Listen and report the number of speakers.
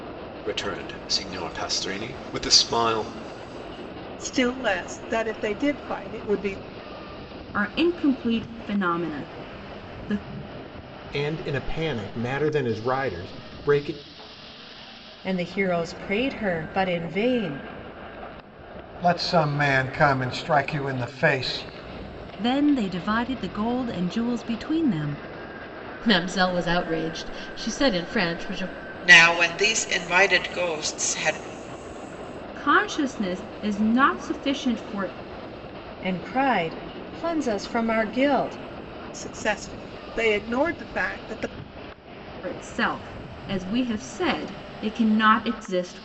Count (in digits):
9